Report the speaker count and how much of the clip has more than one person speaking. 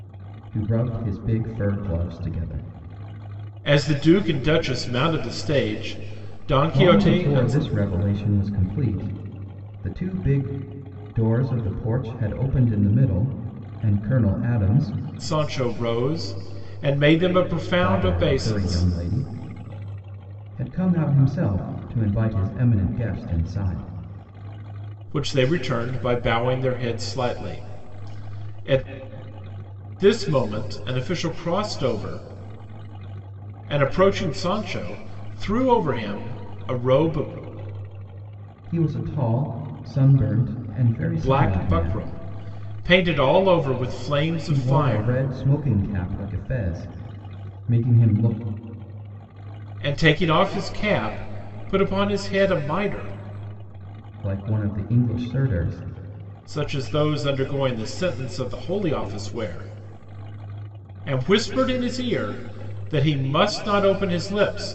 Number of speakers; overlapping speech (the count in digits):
2, about 6%